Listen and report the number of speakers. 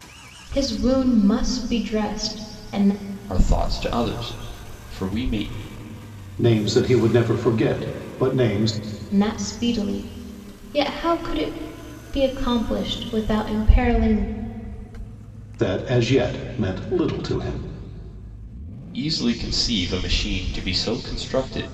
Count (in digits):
3